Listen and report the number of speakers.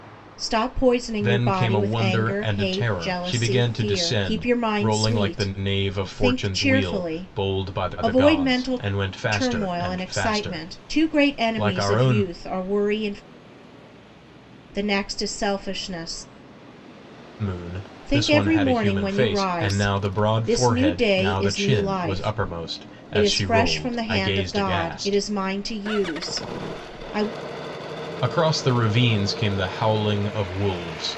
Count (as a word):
two